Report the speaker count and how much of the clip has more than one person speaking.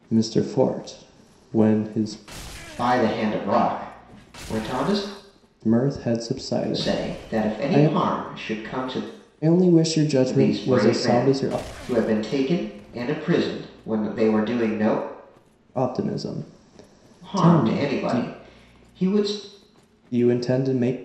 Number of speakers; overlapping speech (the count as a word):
two, about 17%